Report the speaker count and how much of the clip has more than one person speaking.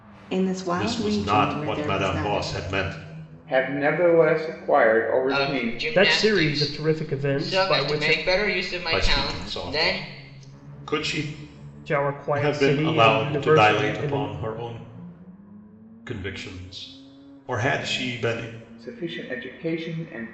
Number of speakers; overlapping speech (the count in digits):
5, about 38%